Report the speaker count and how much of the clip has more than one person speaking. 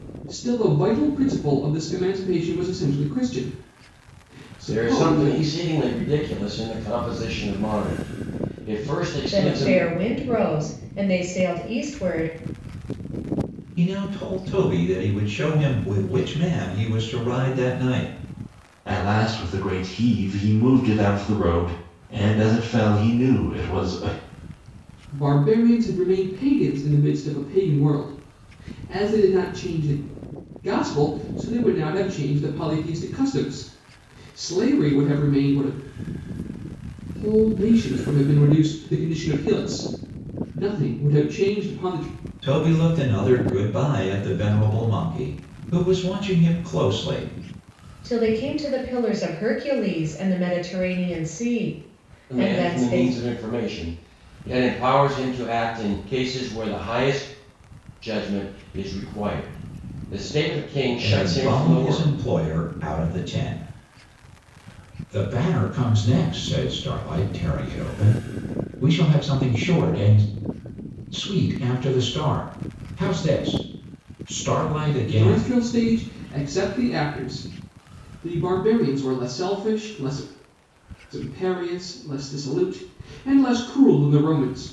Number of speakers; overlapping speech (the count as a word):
five, about 5%